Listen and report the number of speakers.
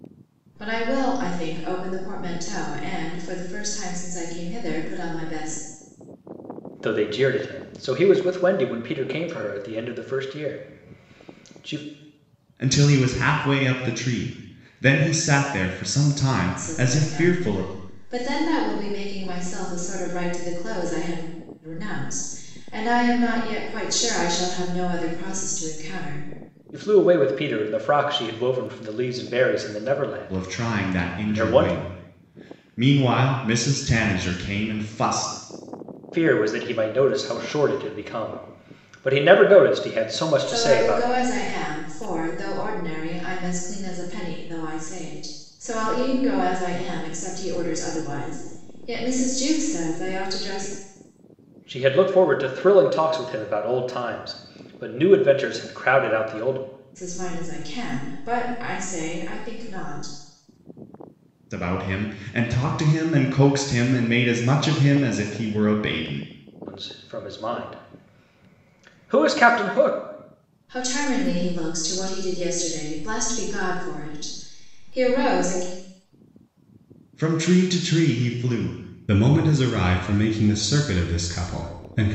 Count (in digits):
3